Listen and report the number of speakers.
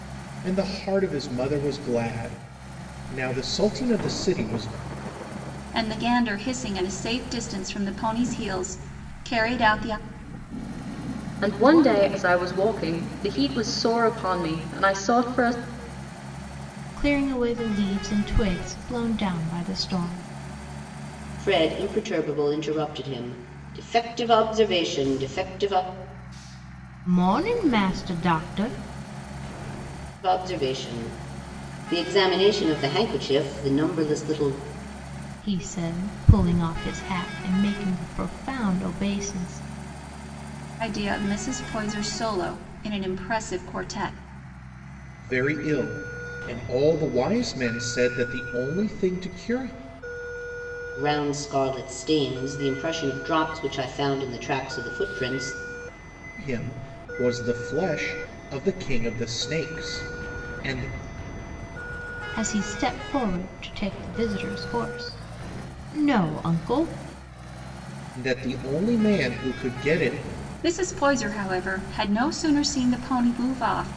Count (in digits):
5